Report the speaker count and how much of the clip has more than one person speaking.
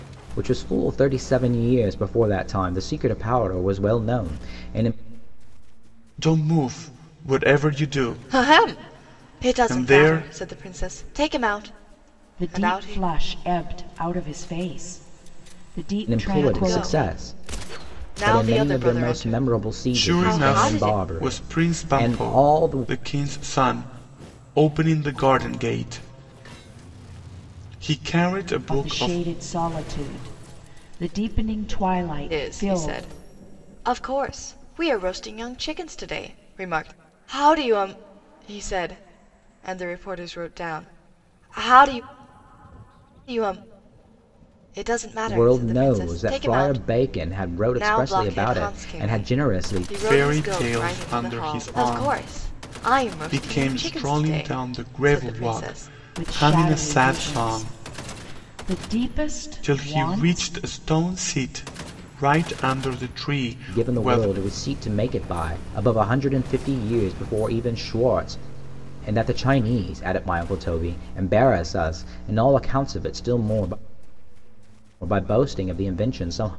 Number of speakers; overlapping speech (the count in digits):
4, about 29%